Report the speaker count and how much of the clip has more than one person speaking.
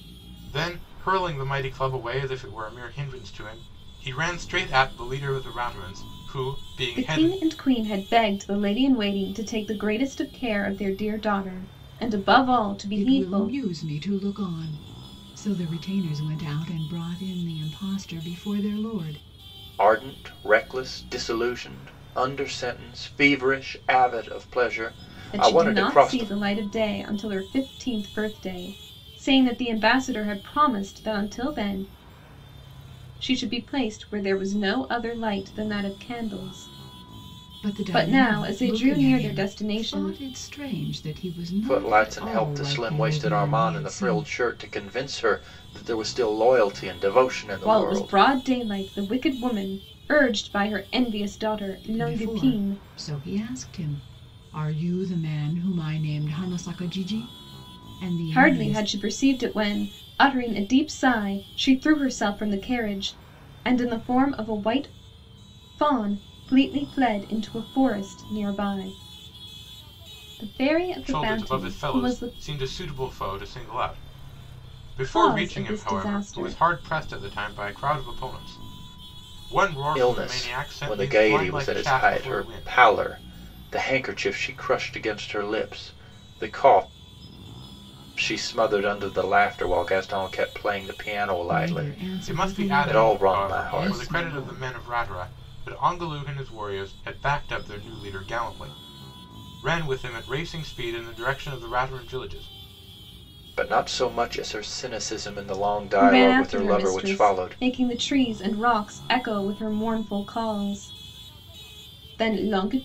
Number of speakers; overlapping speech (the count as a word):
four, about 18%